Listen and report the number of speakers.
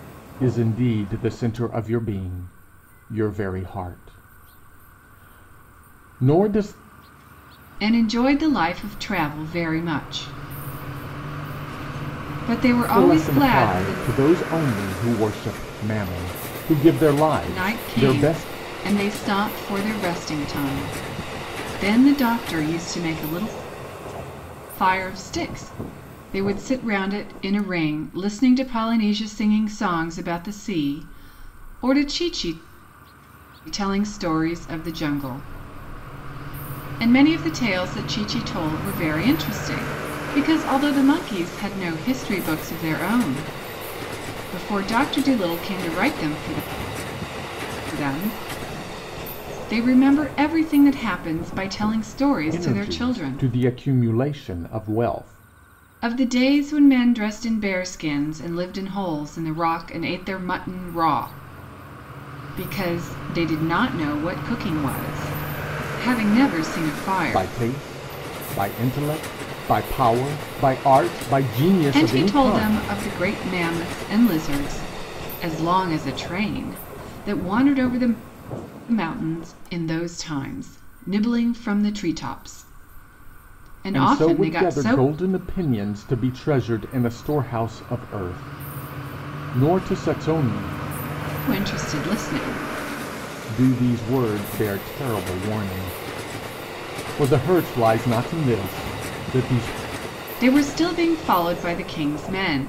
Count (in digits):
2